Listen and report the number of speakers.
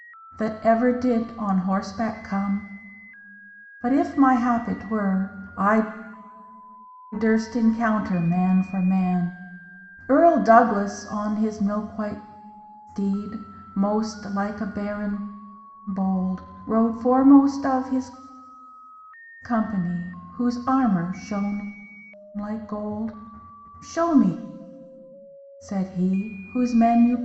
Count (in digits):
1